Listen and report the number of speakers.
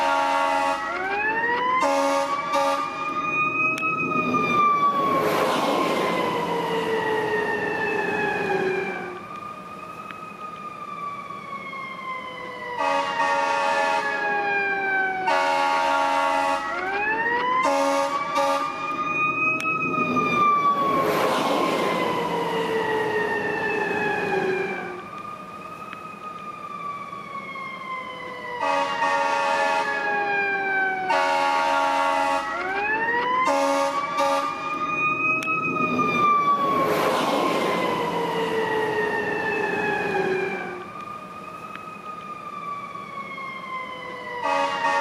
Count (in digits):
0